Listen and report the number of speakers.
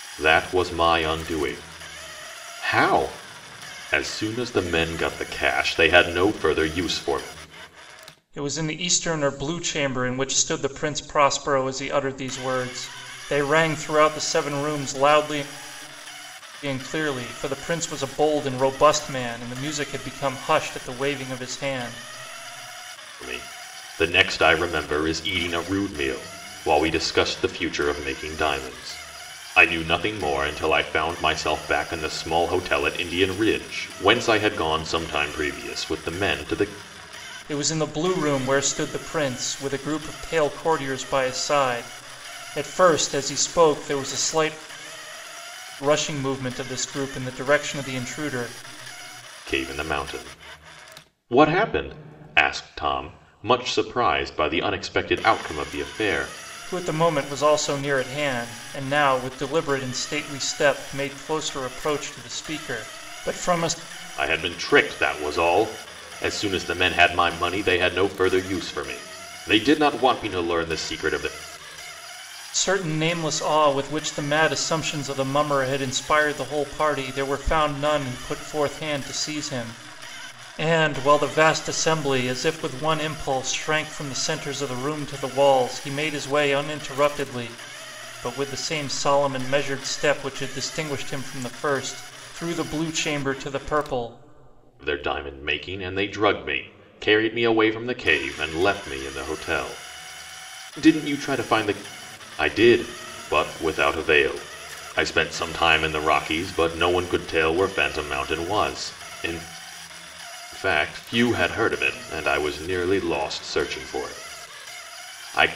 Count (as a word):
two